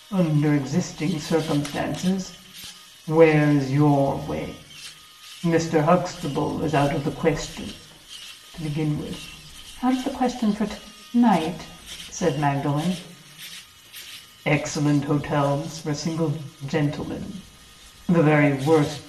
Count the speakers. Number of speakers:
one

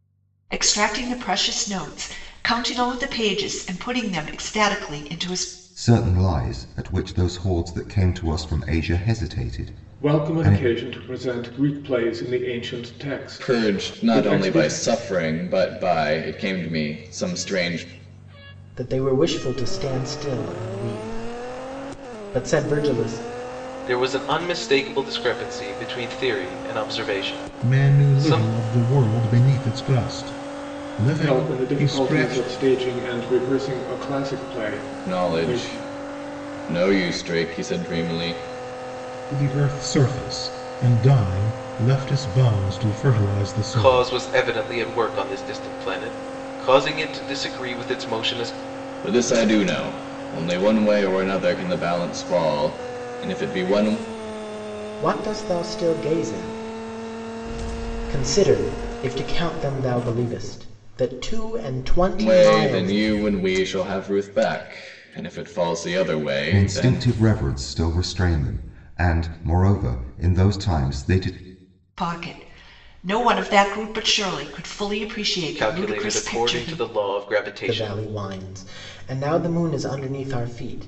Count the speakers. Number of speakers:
seven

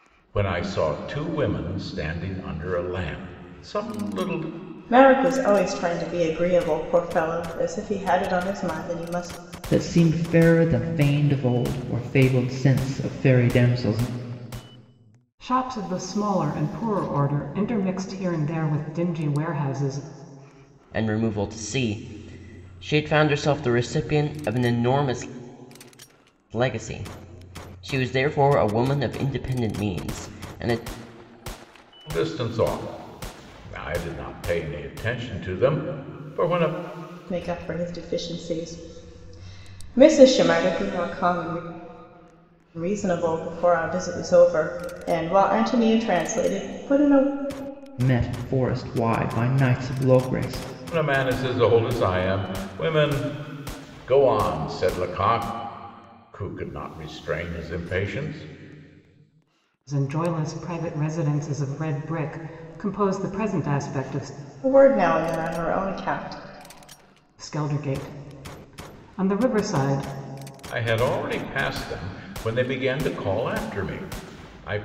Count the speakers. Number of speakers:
five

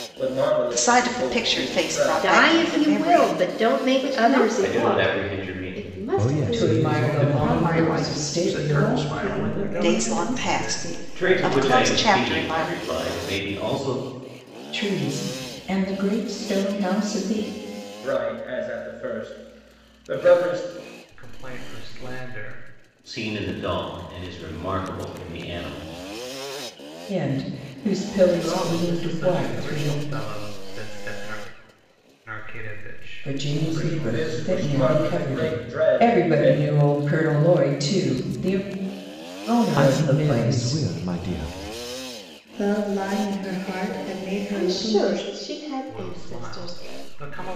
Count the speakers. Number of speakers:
ten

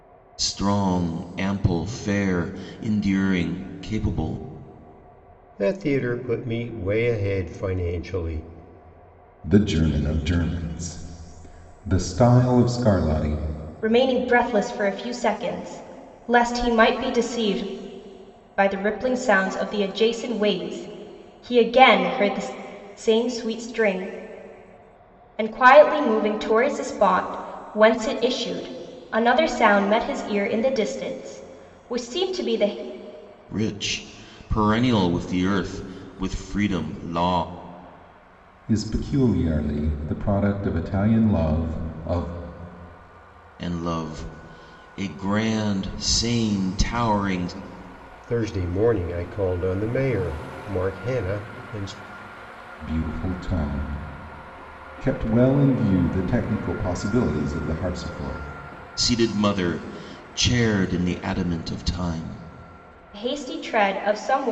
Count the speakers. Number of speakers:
four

